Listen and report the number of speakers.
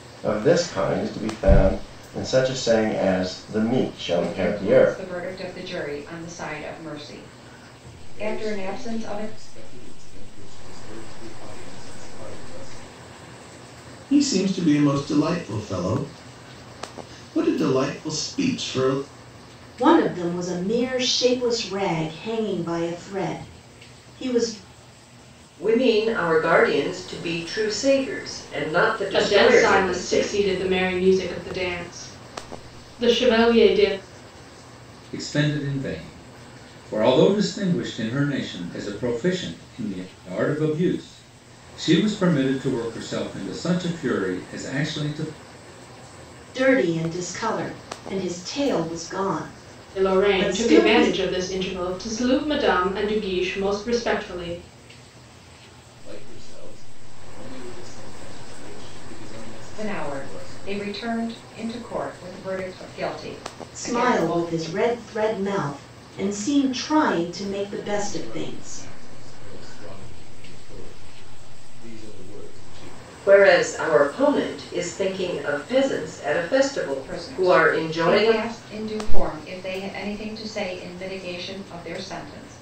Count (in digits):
8